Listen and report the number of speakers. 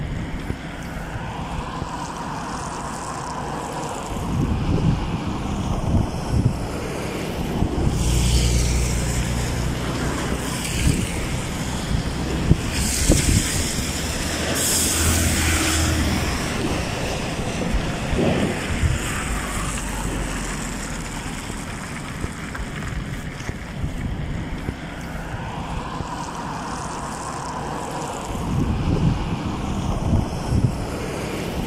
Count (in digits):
0